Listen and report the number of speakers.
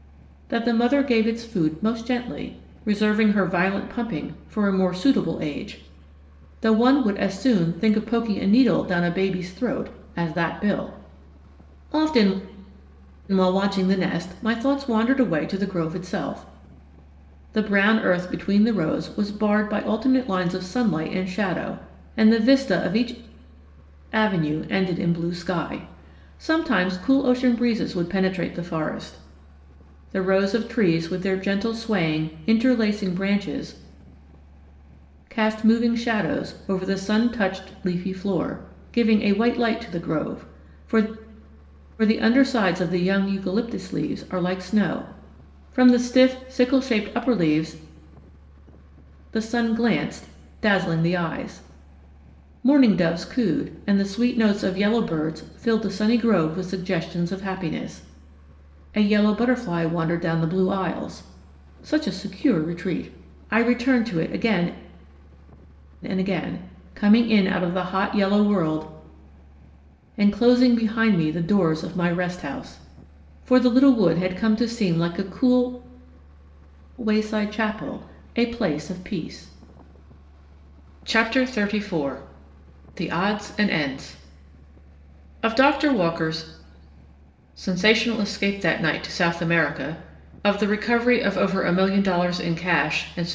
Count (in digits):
1